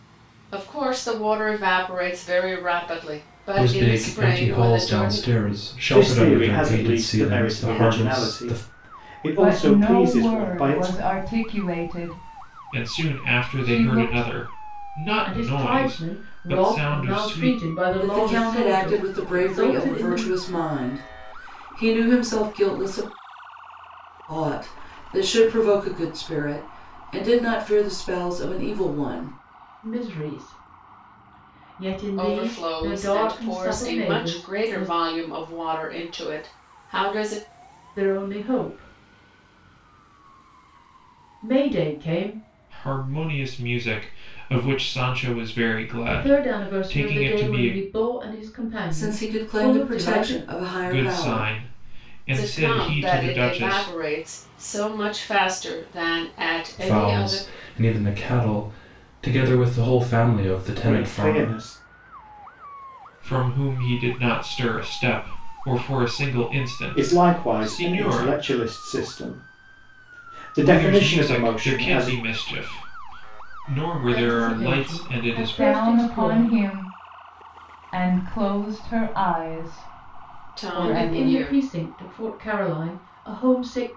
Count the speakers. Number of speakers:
seven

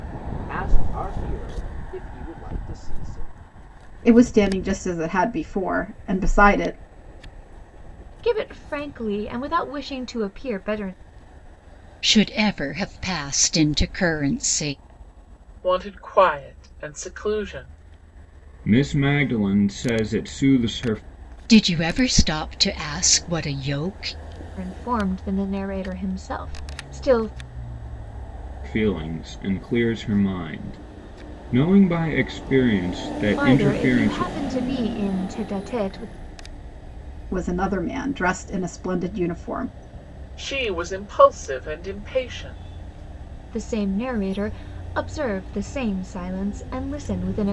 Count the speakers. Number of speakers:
six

